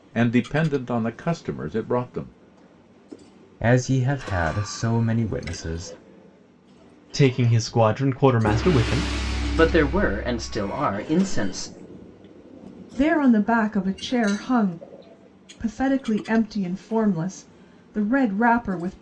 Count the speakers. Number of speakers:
5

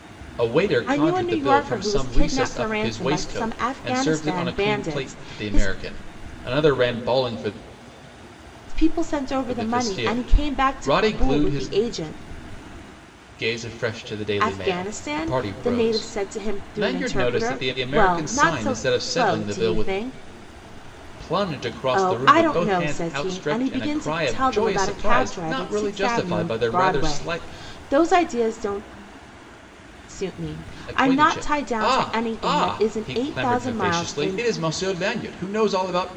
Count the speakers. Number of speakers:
2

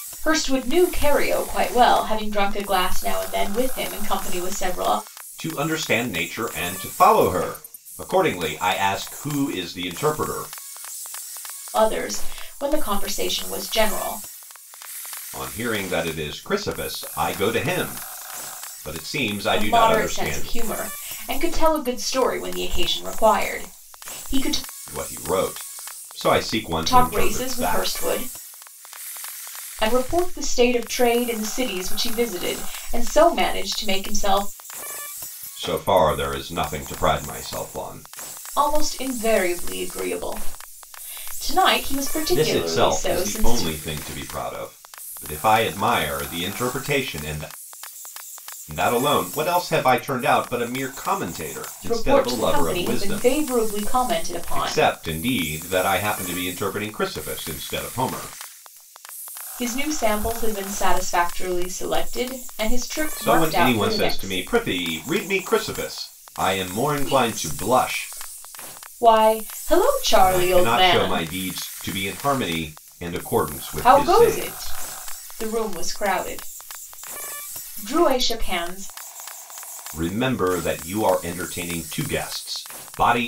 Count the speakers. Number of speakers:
2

